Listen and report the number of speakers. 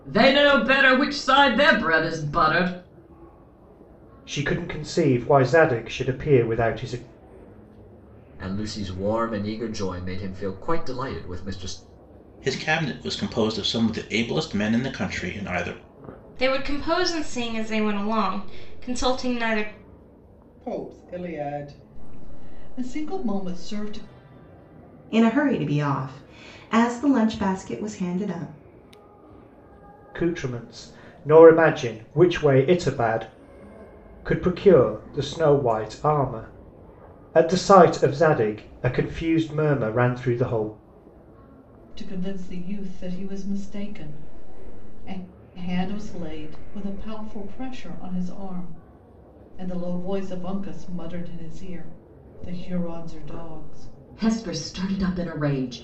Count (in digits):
7